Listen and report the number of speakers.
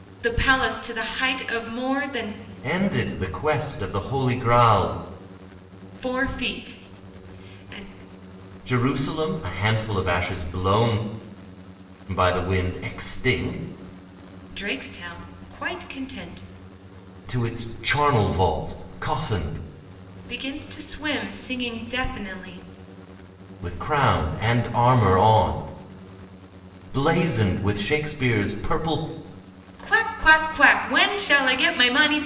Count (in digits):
2